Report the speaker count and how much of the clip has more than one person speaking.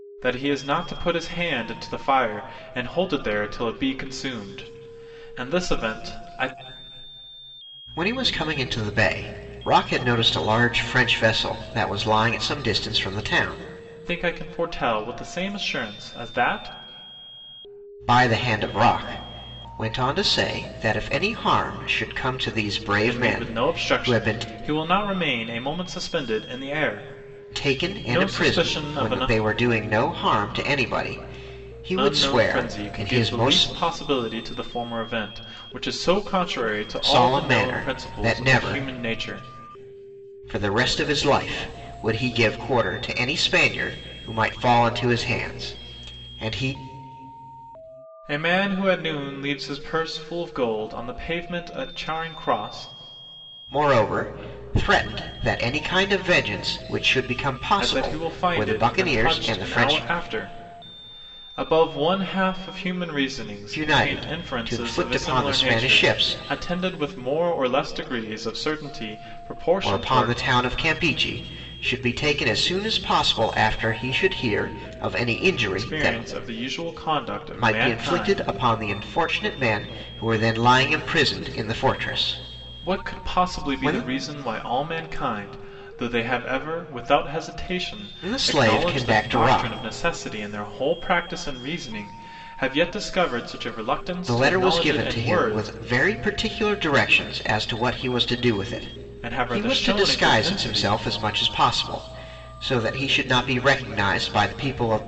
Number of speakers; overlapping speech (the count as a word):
two, about 19%